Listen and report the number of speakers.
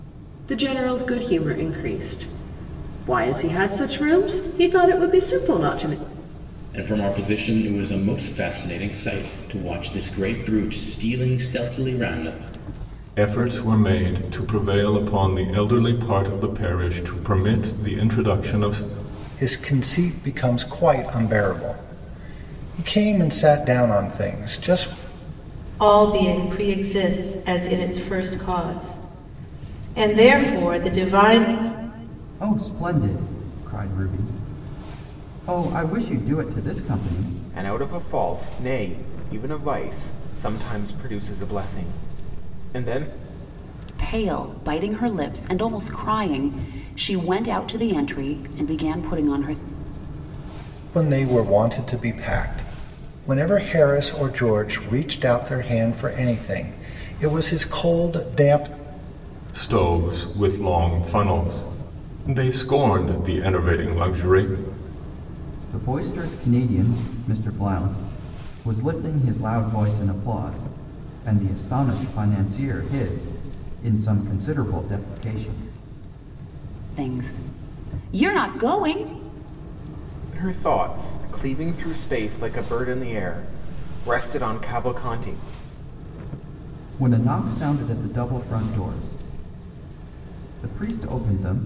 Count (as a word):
eight